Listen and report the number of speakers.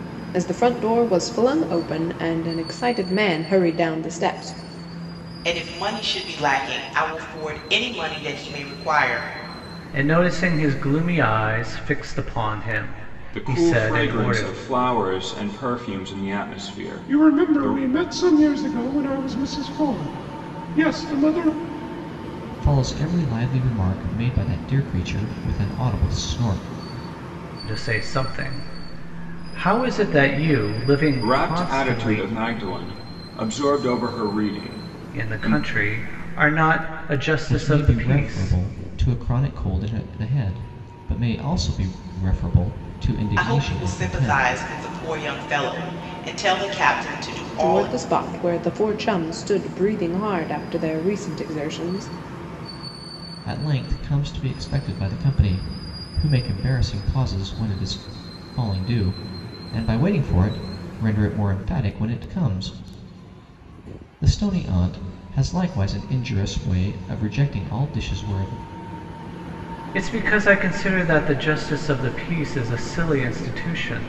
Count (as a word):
six